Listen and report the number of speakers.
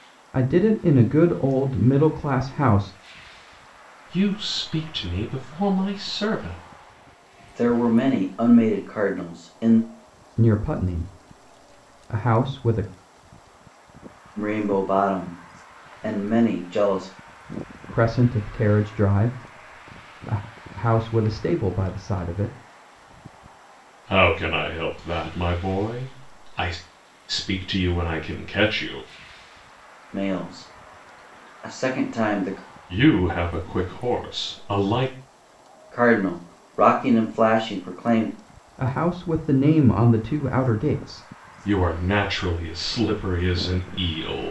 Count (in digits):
3